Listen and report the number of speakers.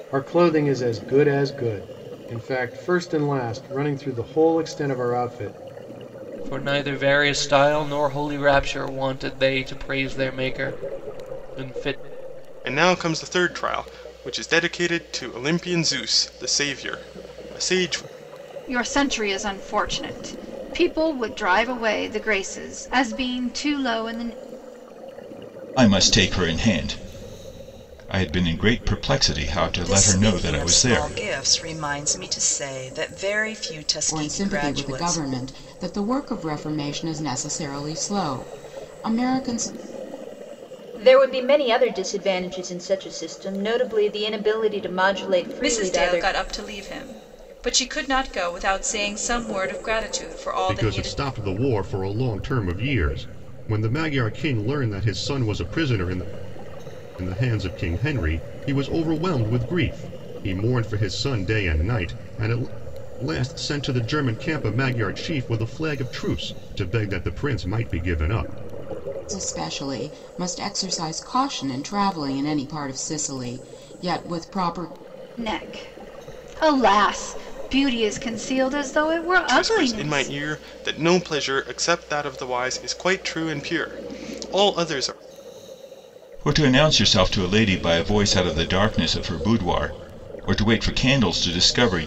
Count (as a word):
ten